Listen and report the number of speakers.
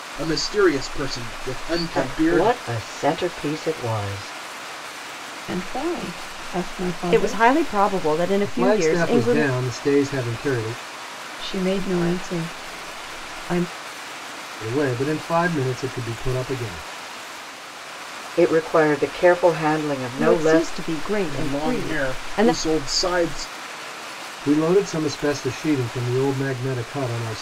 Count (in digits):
5